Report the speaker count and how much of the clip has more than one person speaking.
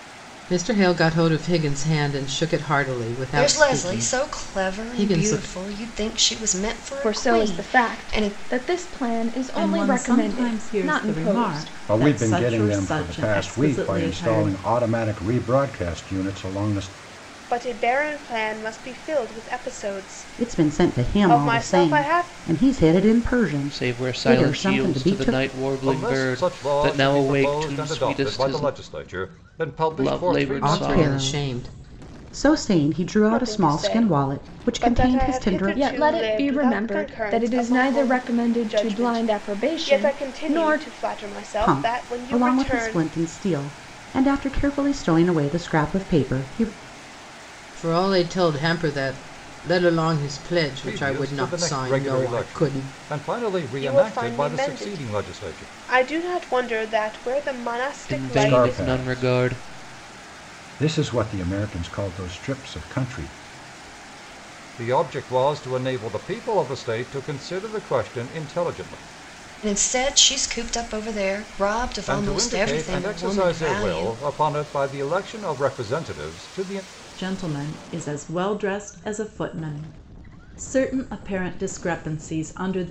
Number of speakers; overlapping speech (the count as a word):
nine, about 41%